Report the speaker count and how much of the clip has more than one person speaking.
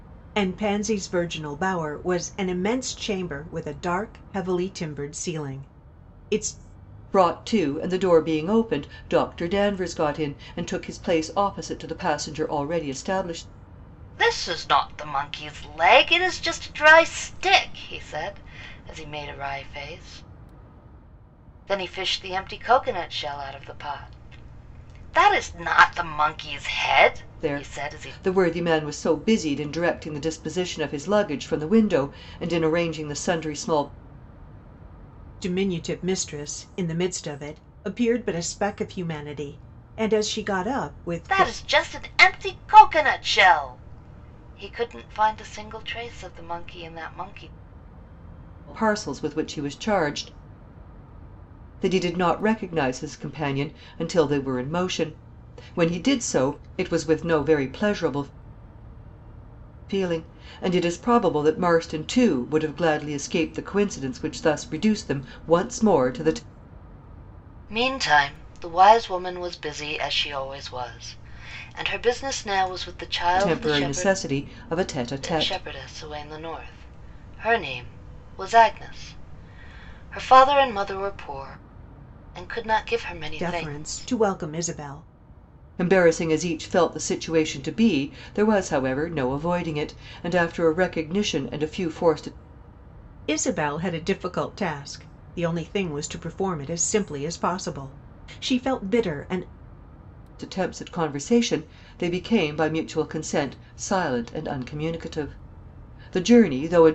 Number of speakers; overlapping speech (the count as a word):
three, about 3%